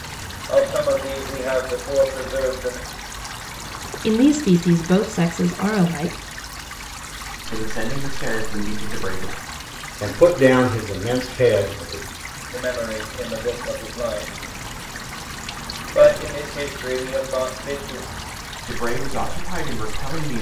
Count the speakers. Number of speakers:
four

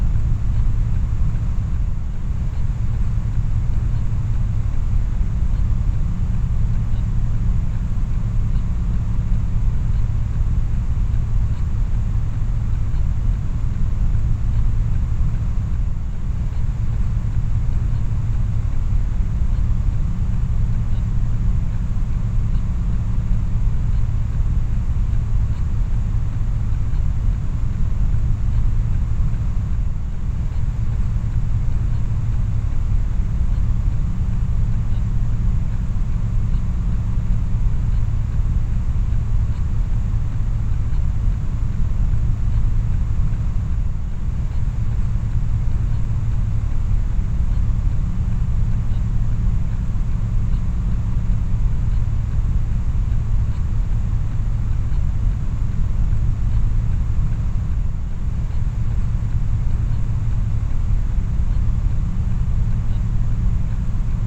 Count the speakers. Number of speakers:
zero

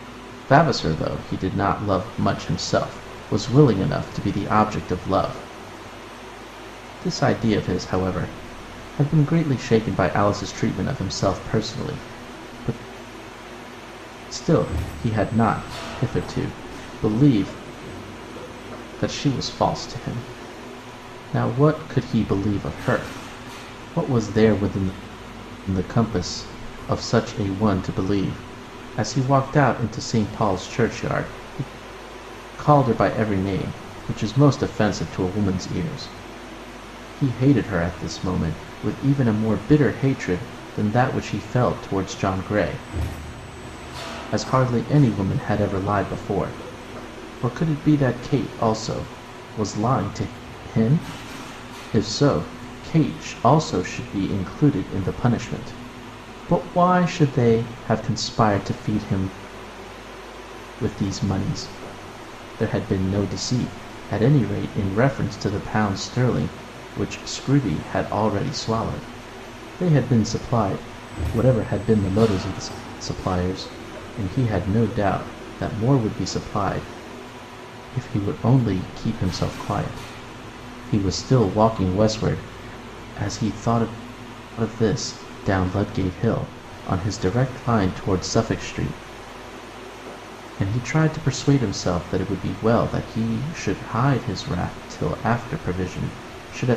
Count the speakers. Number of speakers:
one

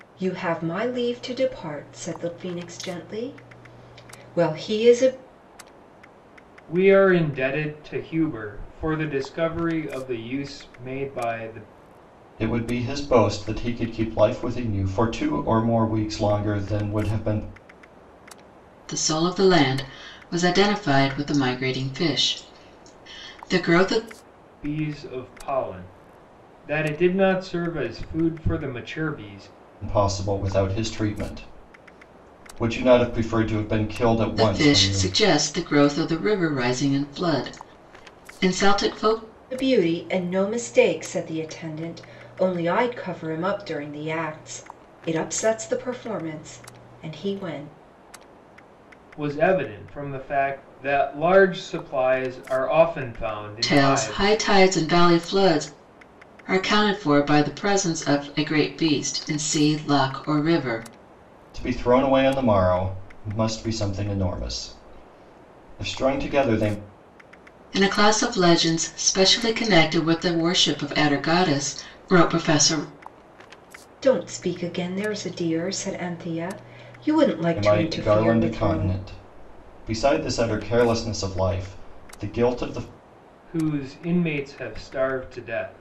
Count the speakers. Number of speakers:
four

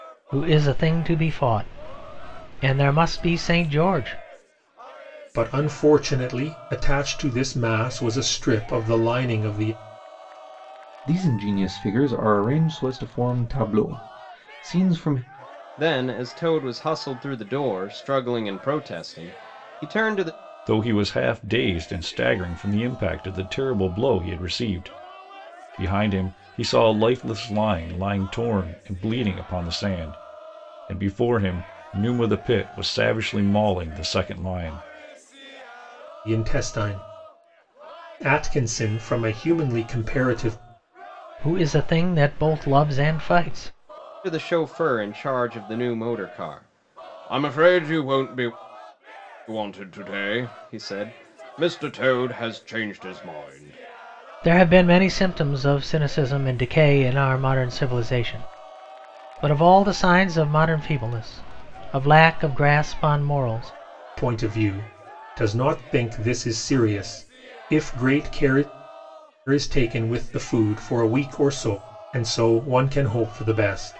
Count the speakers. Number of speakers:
five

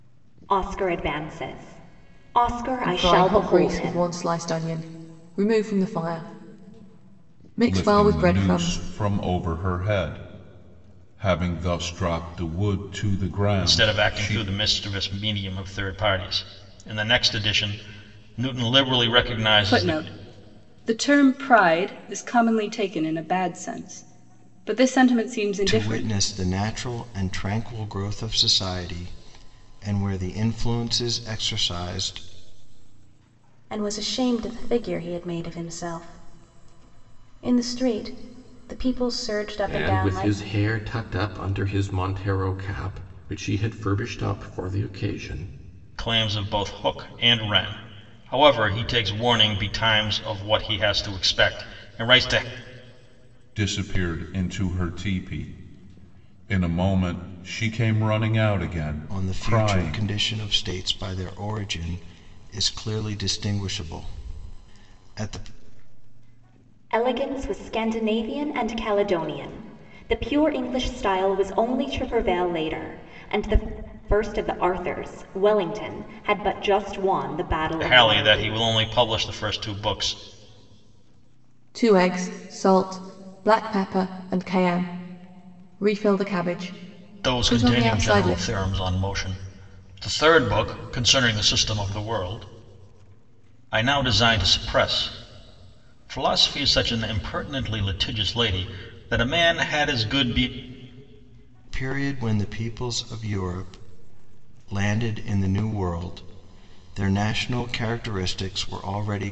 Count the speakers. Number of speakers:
eight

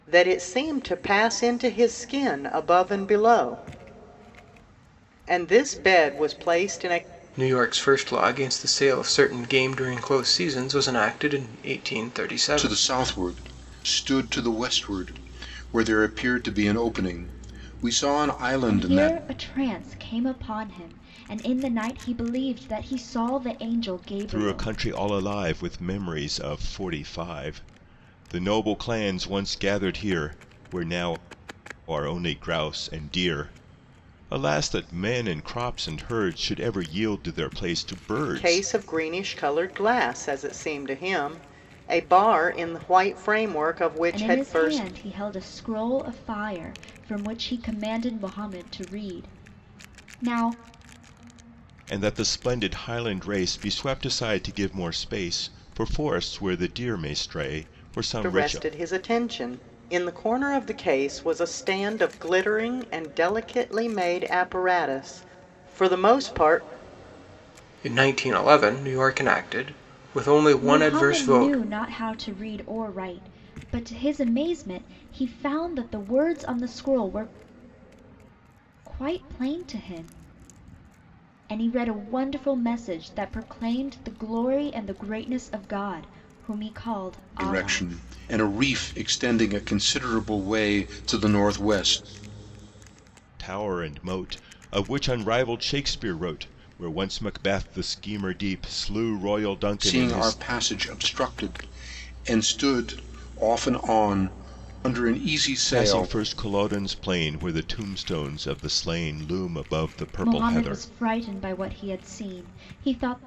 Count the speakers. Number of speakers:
five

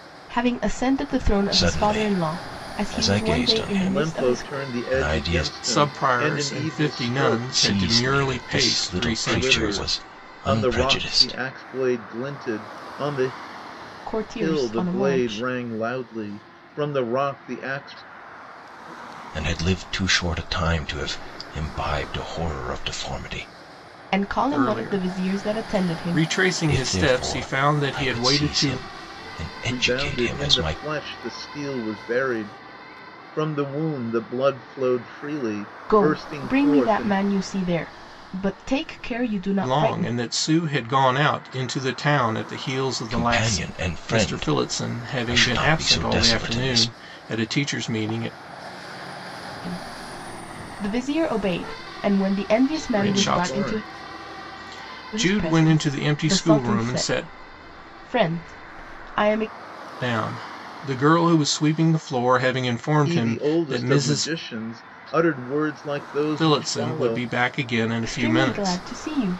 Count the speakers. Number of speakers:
four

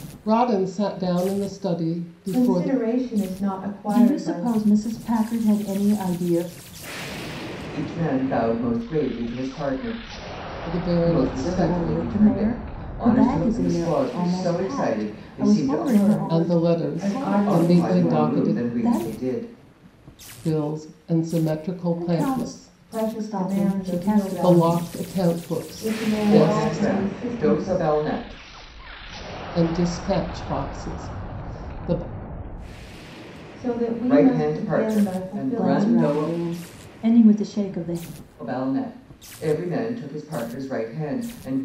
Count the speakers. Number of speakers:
four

